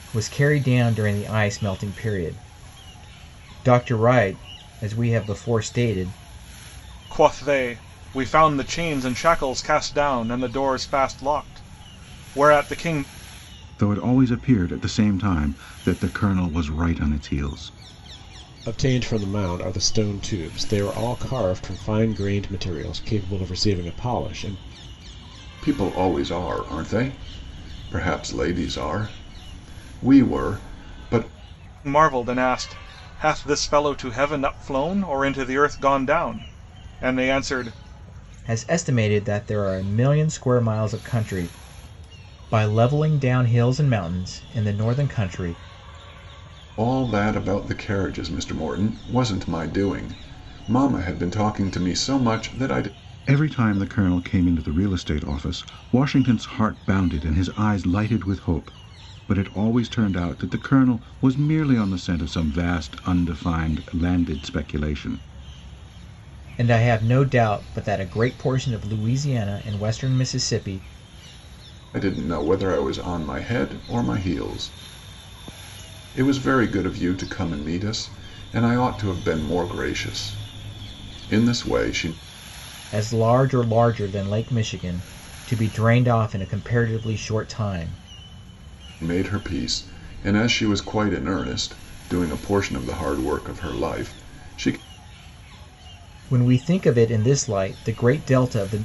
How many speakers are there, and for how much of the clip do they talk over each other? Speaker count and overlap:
five, no overlap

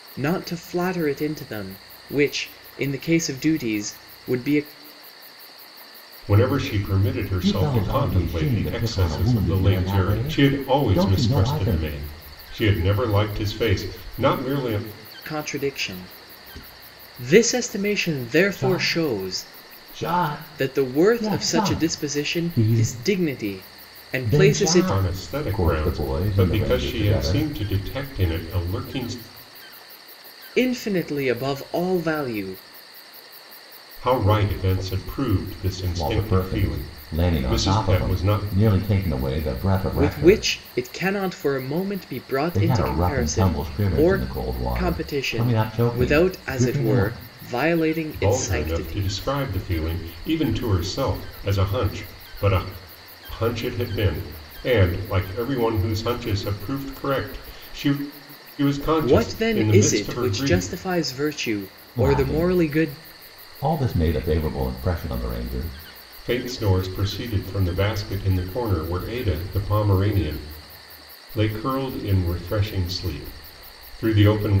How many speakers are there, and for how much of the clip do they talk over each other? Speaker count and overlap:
three, about 30%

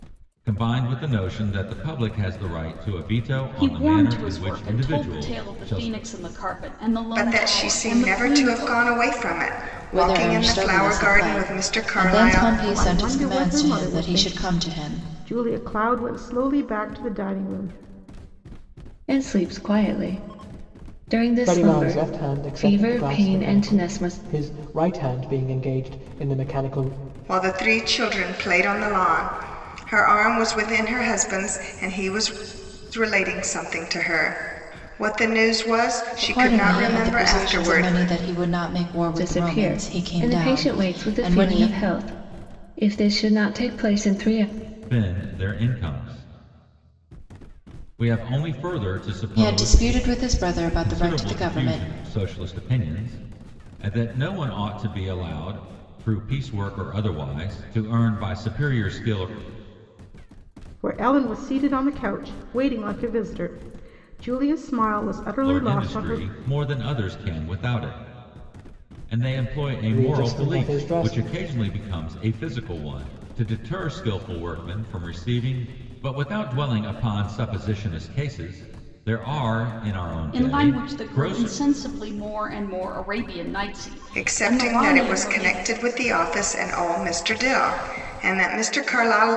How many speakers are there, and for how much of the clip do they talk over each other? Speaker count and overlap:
seven, about 26%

